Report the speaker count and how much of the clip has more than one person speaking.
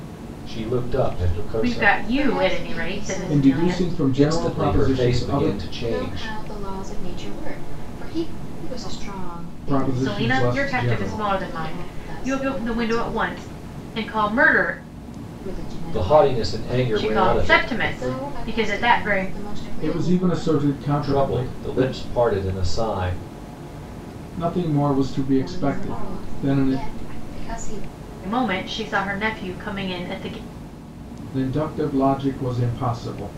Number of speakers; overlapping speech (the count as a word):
five, about 58%